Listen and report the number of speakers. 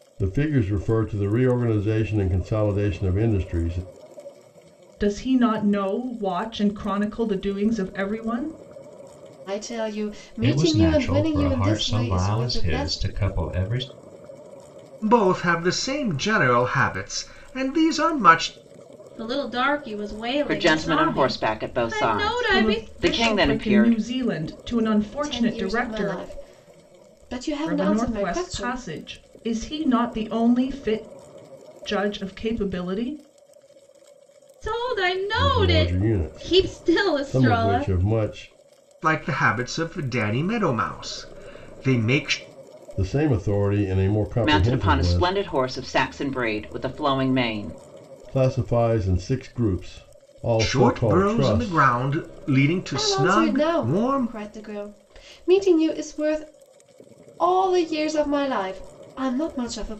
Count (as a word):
seven